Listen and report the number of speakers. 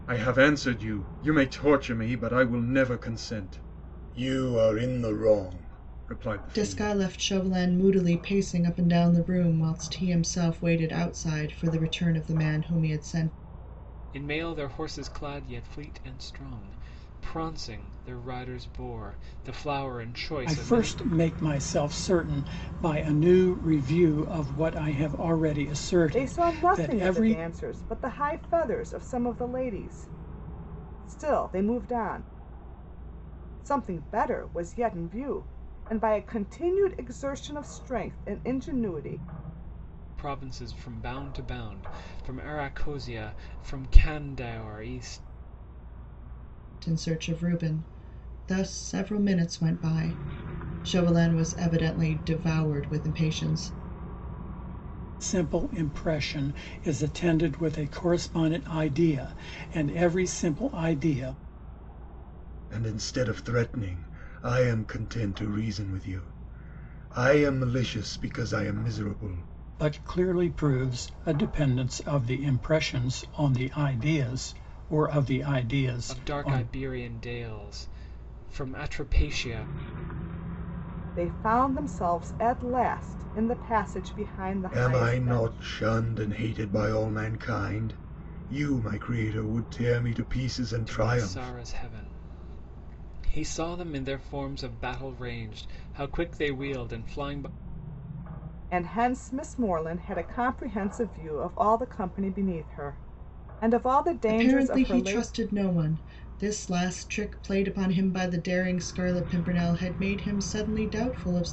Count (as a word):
five